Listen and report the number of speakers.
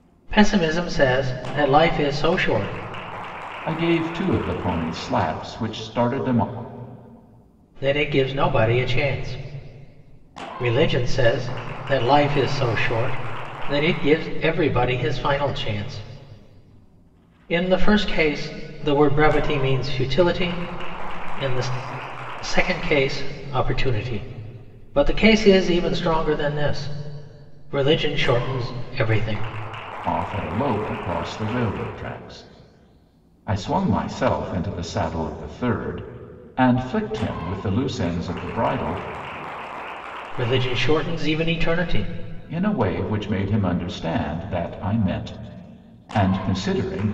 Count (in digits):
2